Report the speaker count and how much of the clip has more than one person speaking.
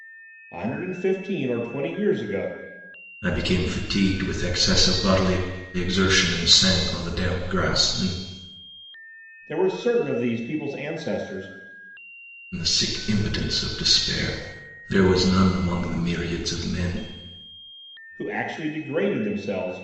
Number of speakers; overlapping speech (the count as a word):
two, no overlap